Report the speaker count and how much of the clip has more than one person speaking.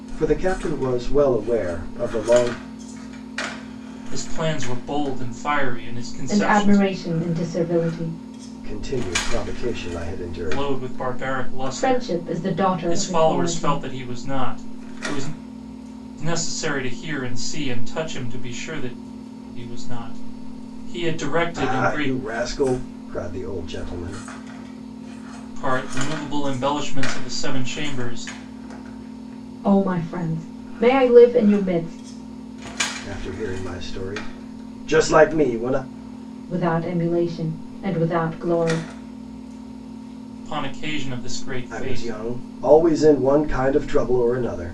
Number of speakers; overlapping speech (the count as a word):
three, about 8%